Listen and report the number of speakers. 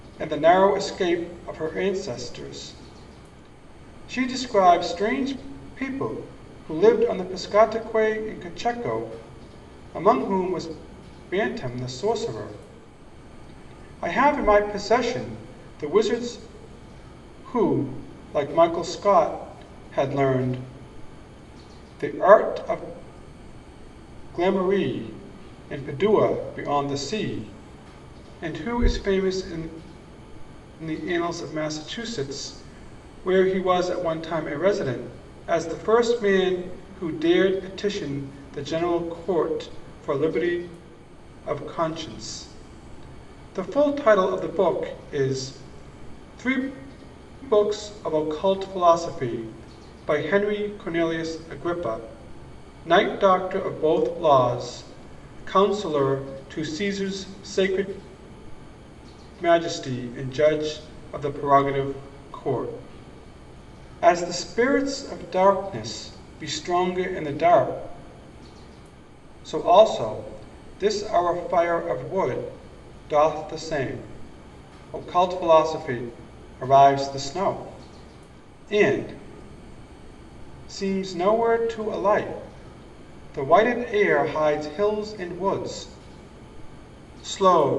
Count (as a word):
one